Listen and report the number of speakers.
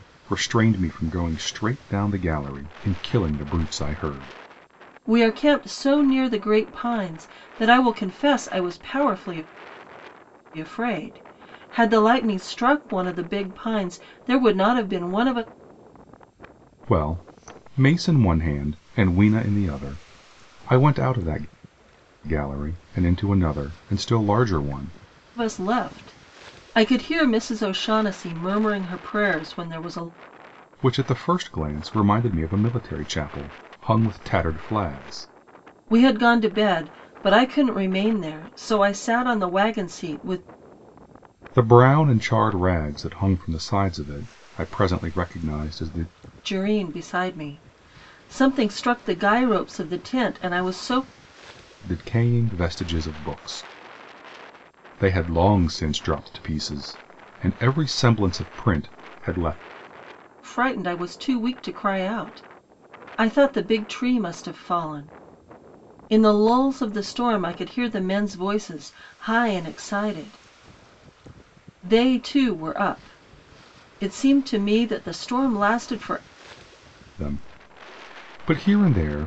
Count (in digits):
2